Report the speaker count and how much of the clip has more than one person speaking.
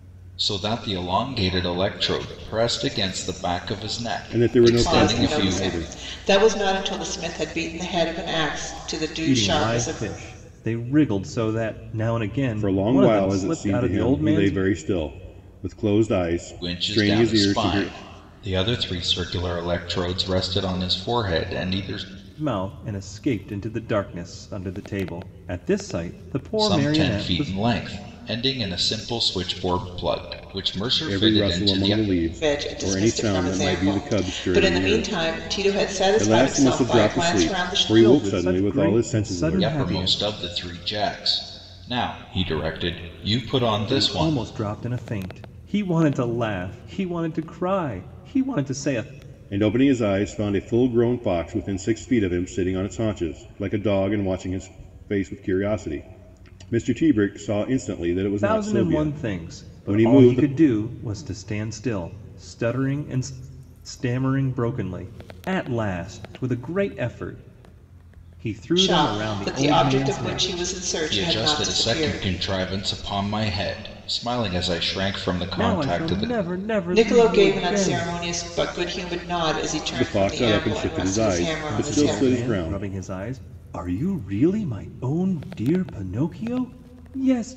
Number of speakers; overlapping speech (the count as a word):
four, about 29%